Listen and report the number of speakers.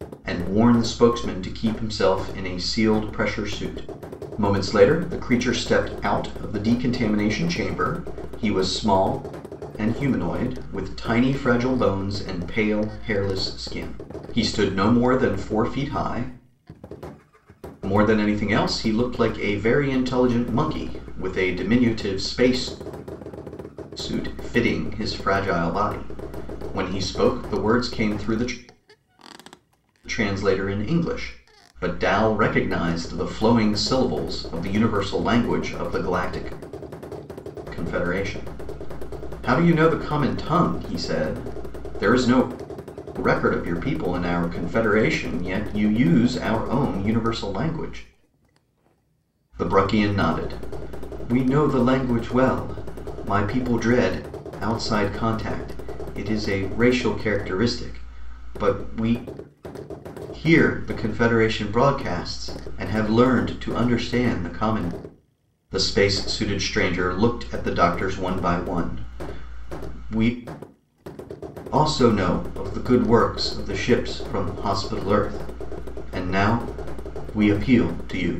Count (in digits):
1